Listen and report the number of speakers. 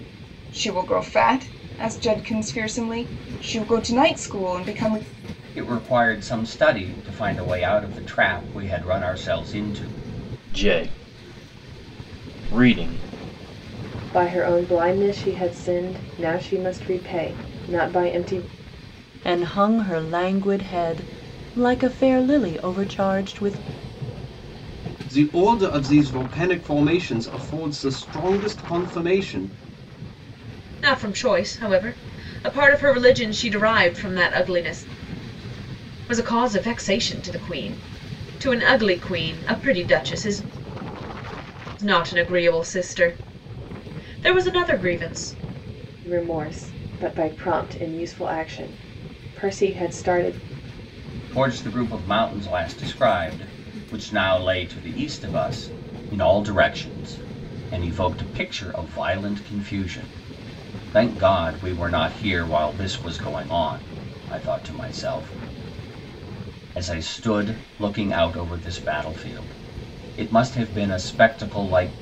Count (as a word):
seven